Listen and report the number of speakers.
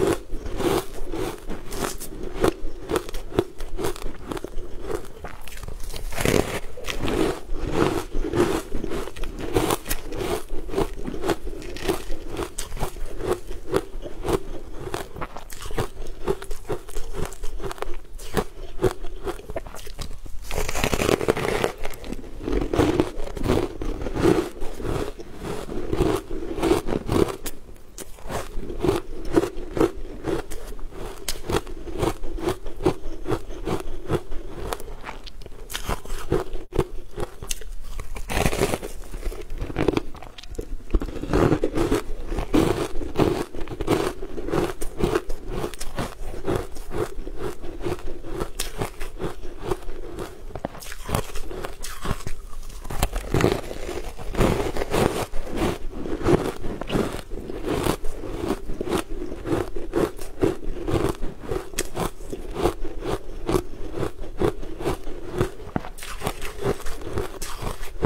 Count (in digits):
0